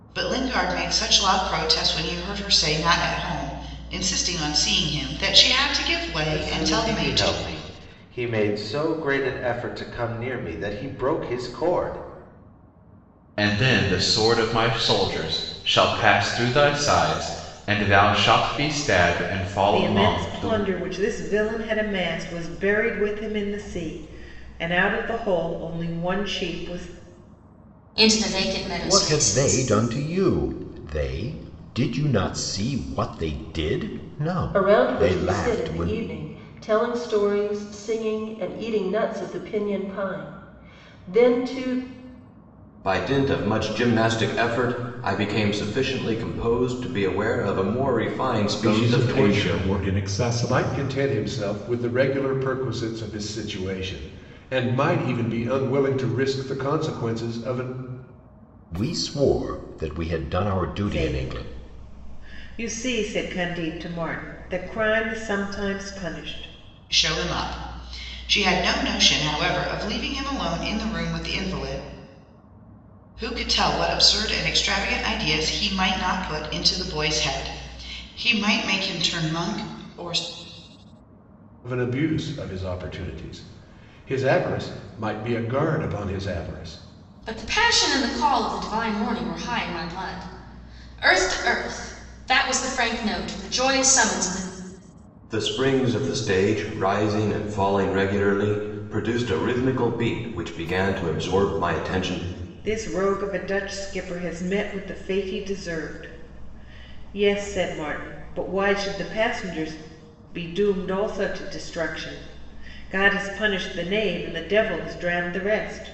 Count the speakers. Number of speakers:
10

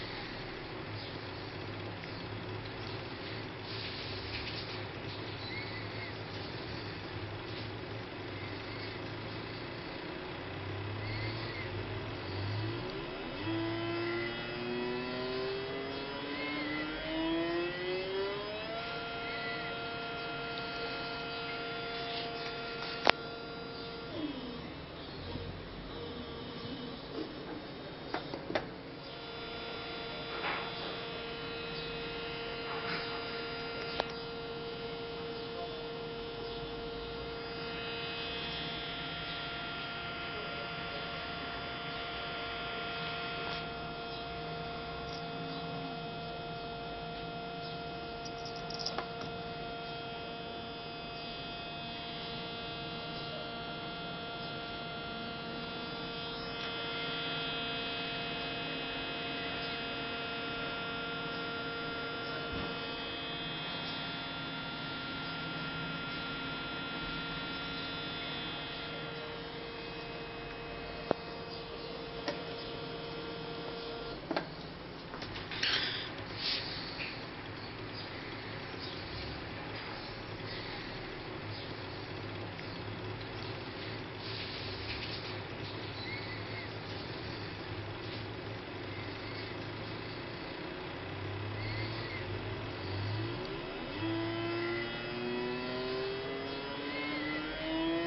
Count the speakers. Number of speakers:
0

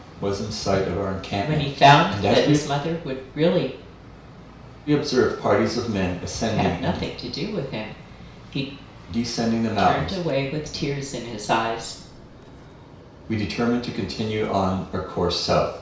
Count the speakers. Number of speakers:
2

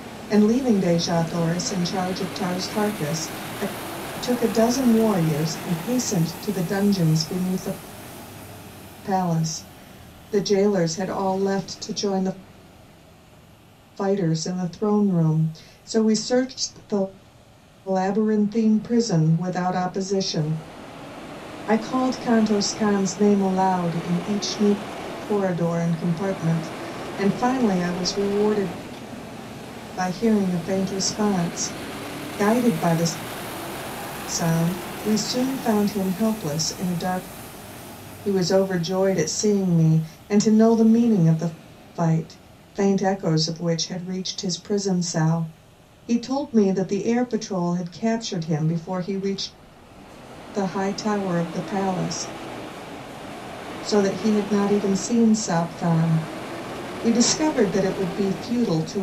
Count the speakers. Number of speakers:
1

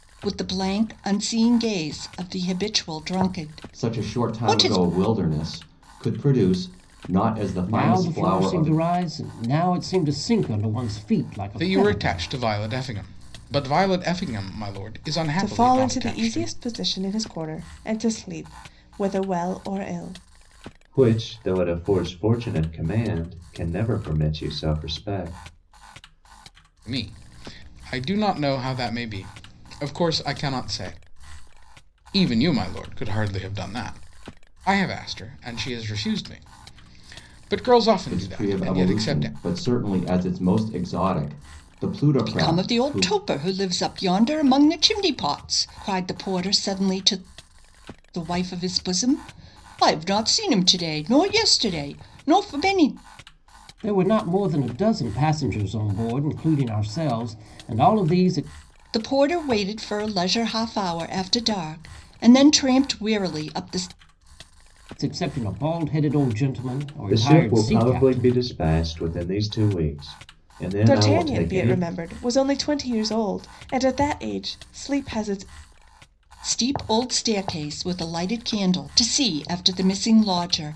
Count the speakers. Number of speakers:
6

